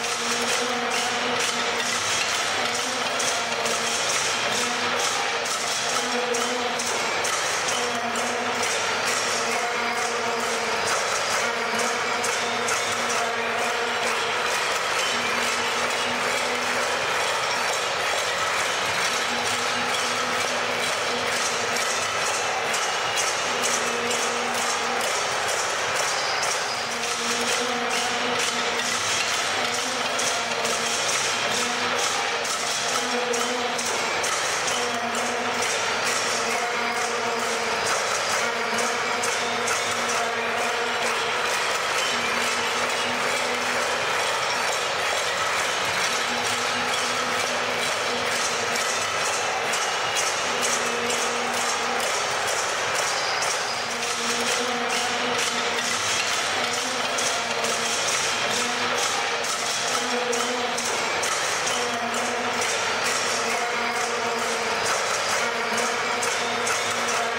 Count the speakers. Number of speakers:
zero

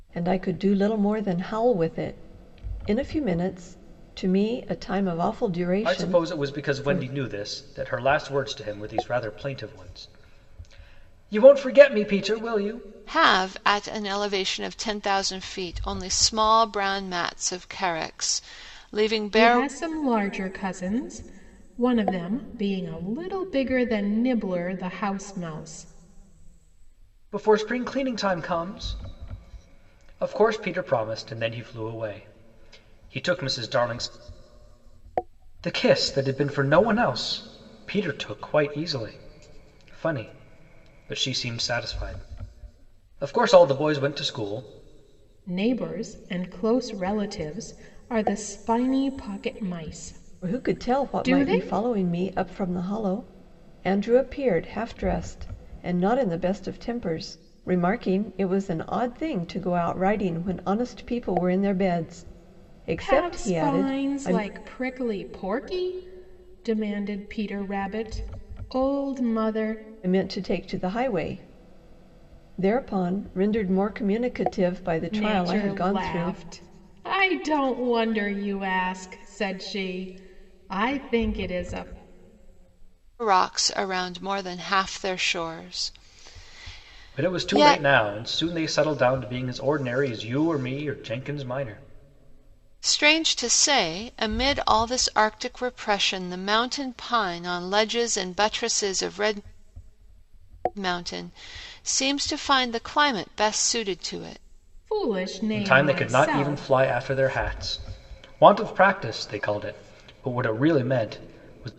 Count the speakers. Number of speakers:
four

